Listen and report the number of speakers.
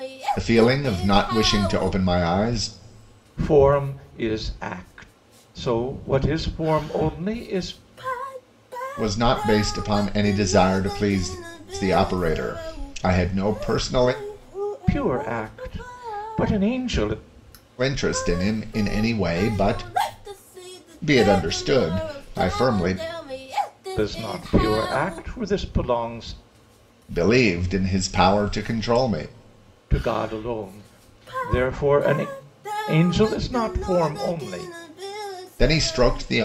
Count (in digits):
2